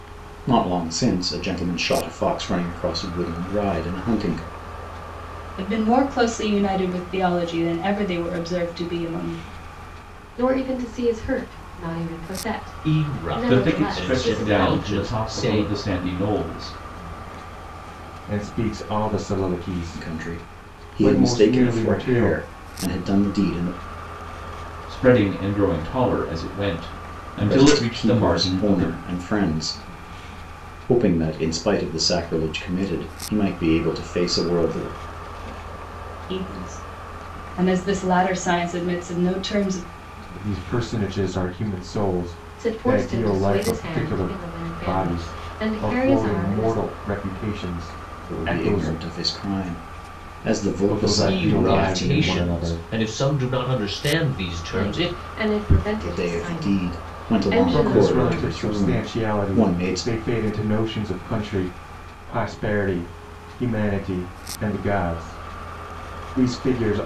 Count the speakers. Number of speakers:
six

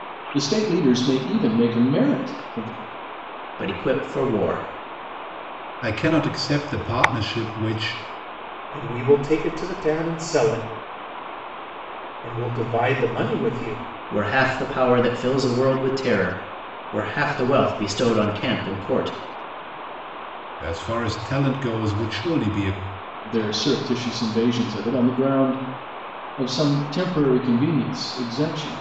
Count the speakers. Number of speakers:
four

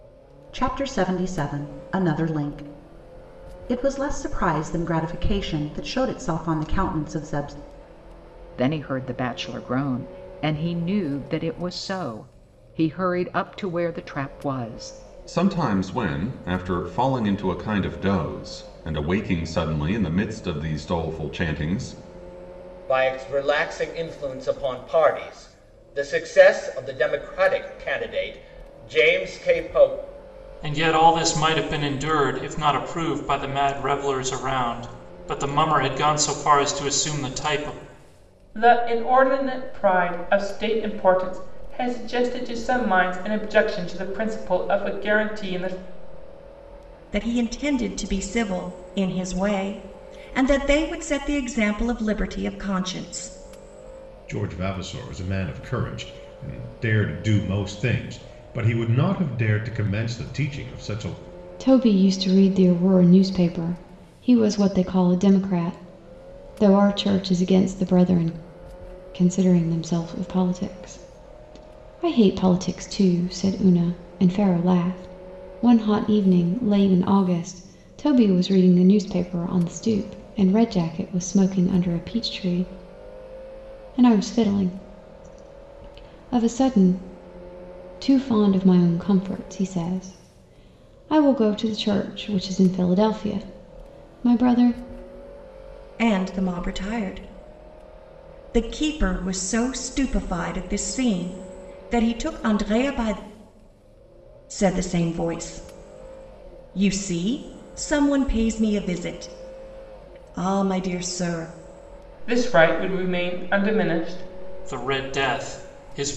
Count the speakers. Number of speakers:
nine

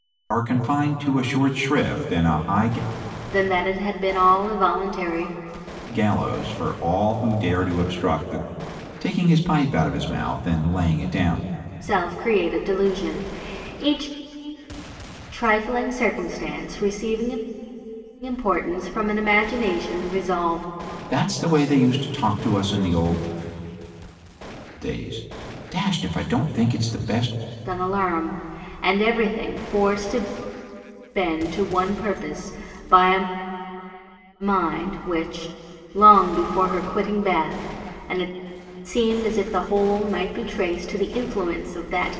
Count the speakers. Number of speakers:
two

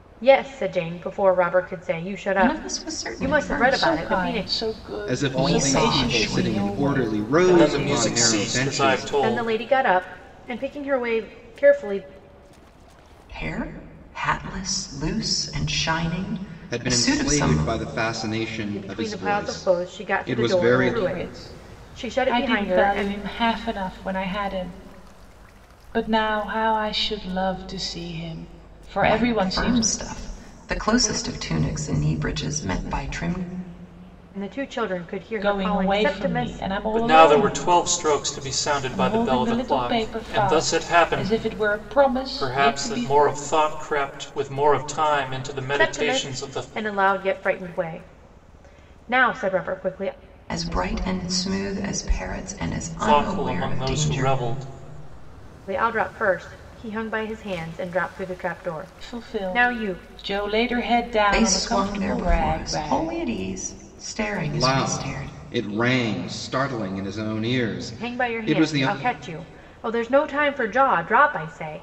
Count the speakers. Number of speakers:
five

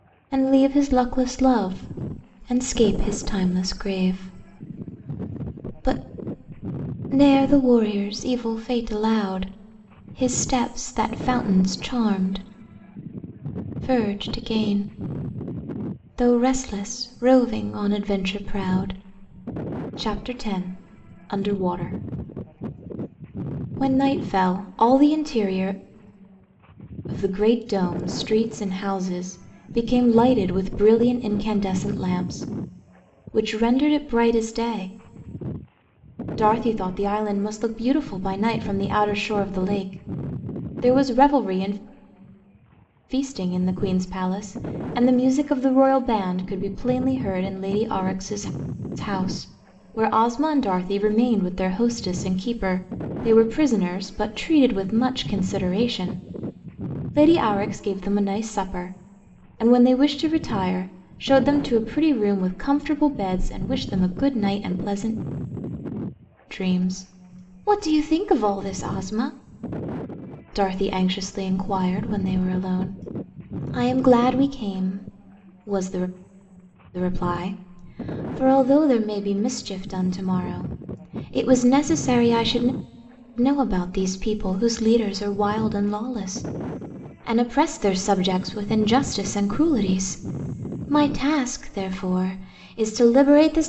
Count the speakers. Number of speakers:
one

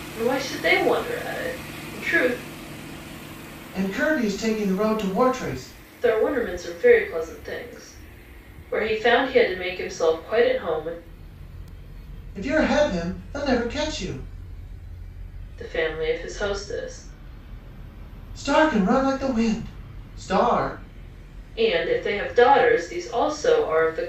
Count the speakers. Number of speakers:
two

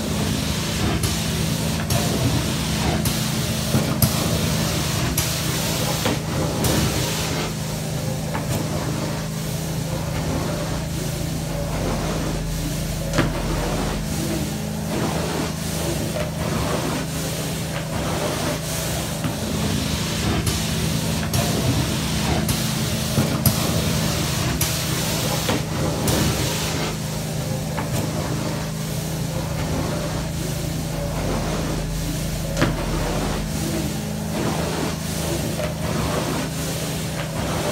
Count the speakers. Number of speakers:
zero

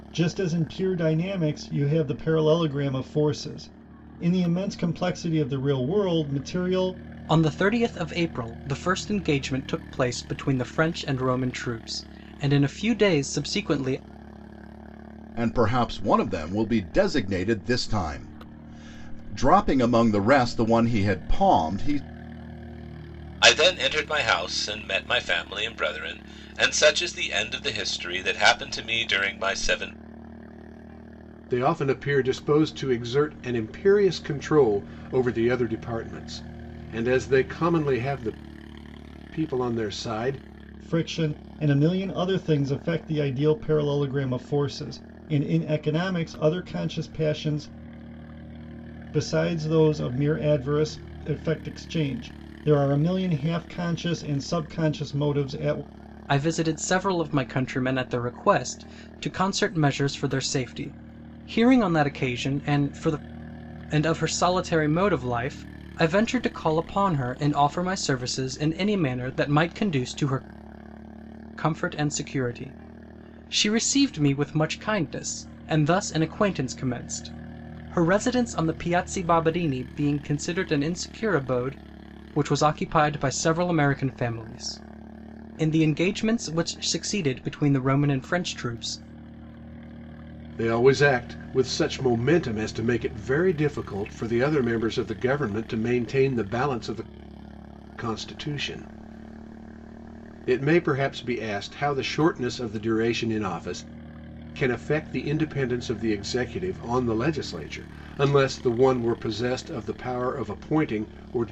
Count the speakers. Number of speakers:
five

